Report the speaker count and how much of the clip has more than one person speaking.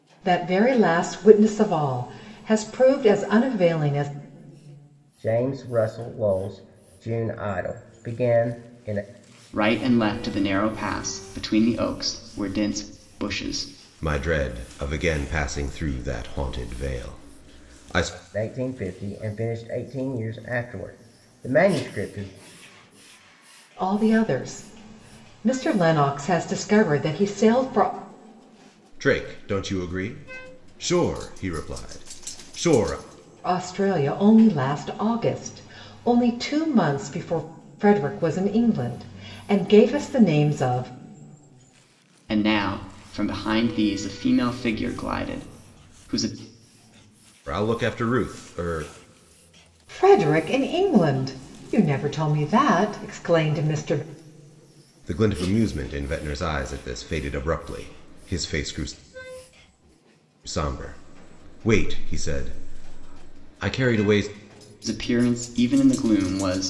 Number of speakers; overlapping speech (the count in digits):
4, no overlap